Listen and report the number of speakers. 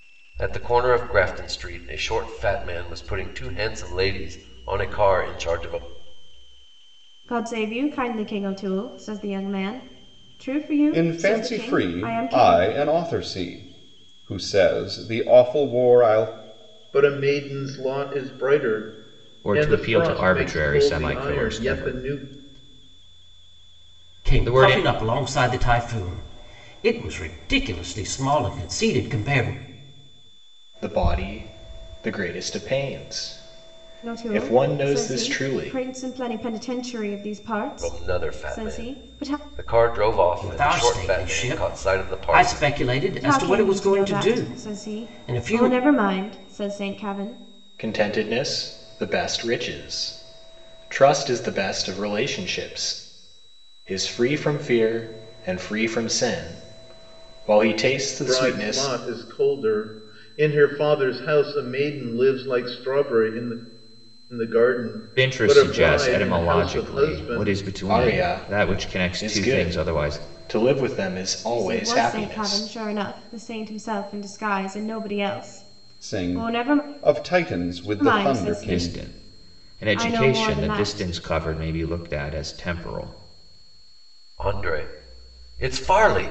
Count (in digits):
7